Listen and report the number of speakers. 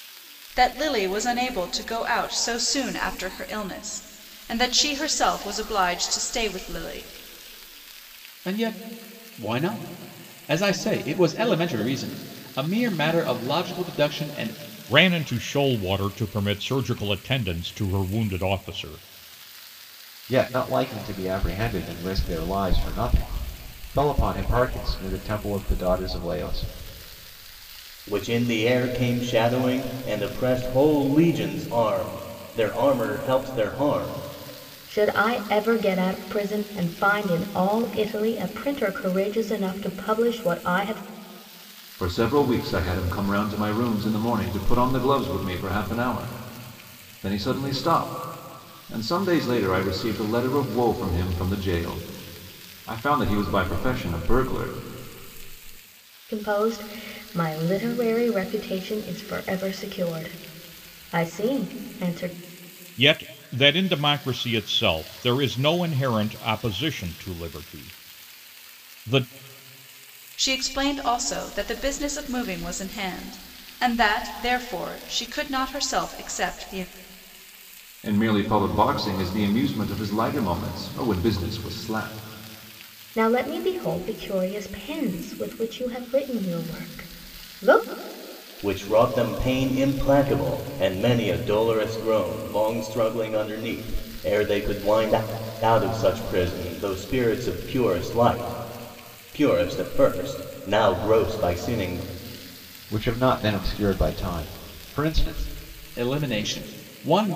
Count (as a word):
seven